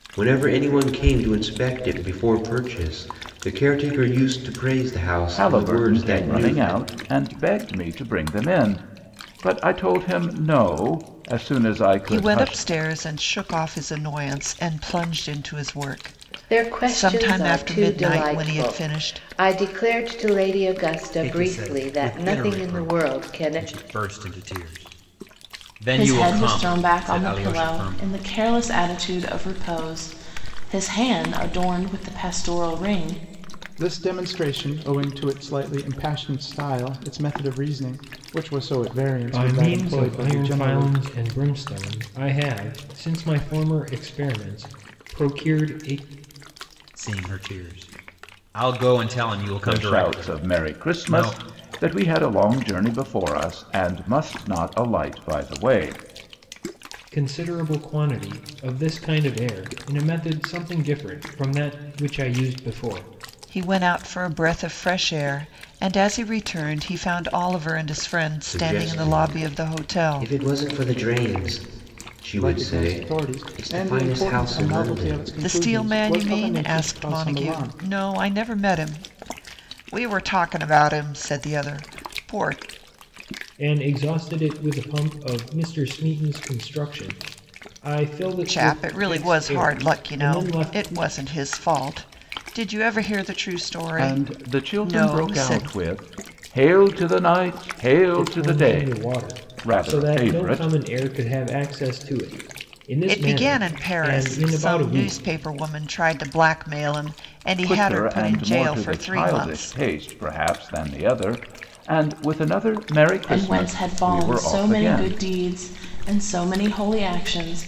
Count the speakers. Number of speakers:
8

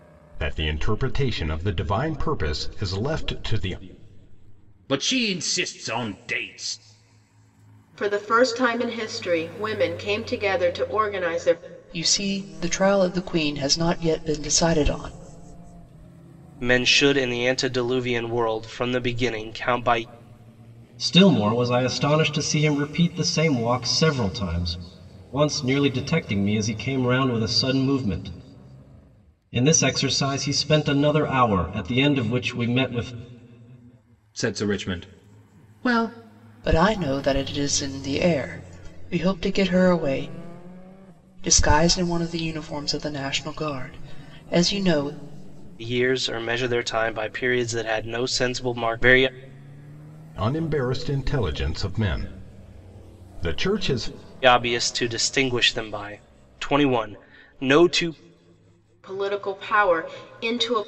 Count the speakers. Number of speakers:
6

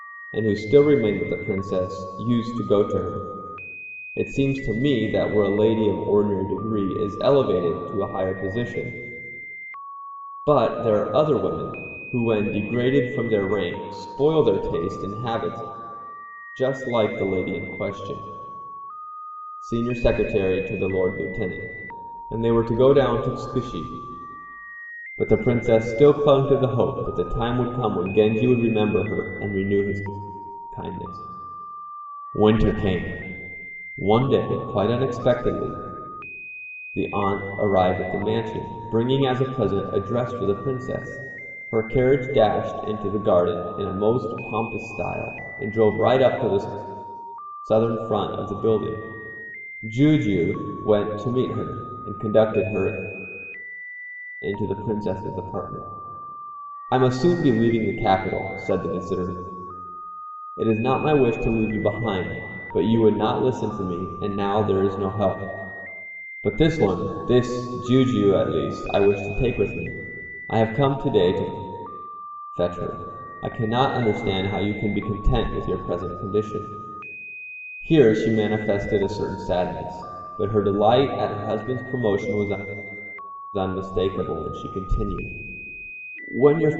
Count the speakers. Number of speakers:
1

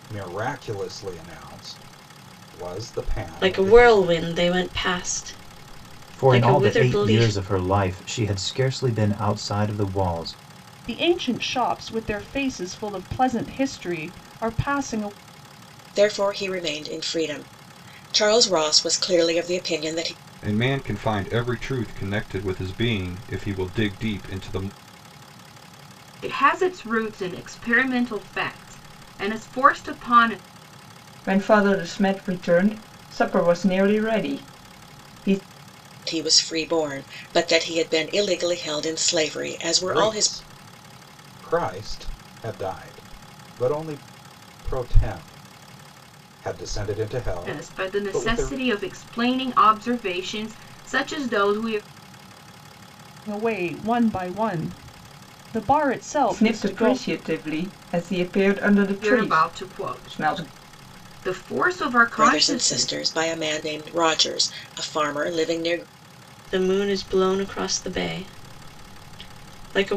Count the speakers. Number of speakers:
8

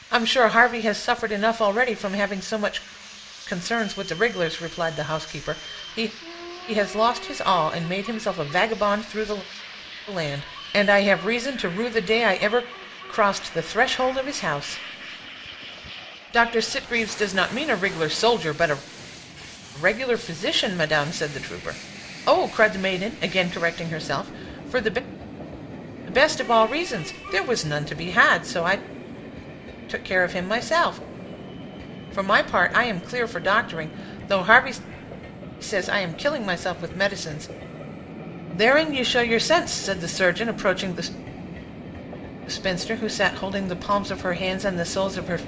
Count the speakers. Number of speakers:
1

